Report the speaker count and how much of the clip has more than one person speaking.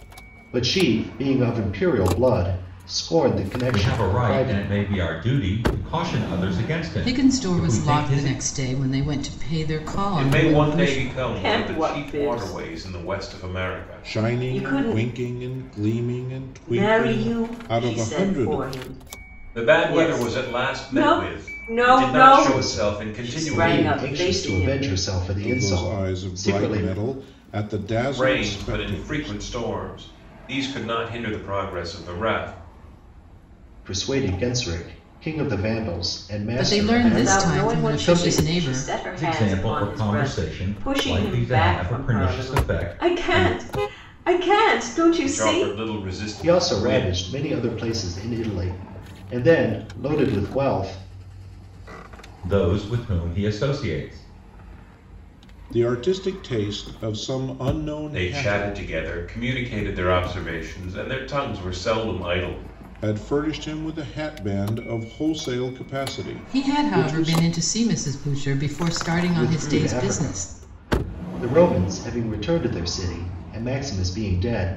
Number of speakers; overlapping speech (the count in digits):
6, about 37%